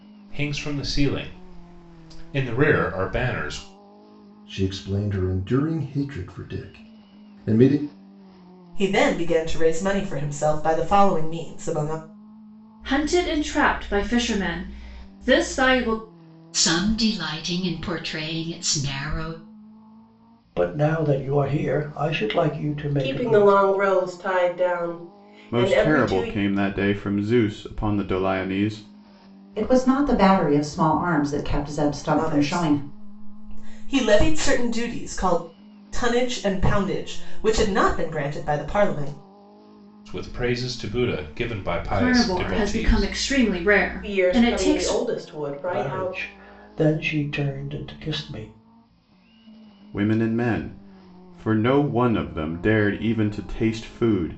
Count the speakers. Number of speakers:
9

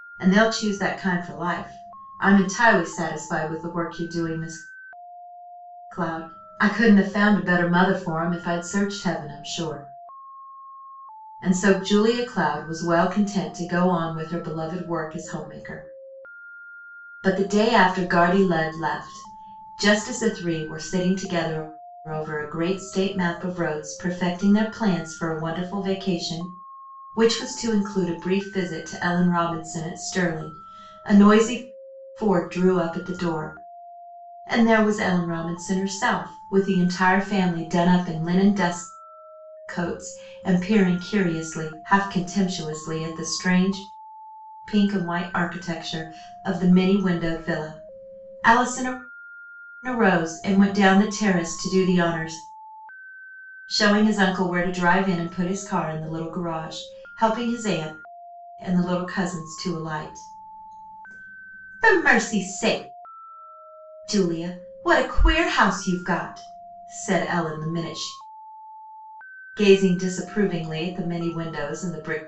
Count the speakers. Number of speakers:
1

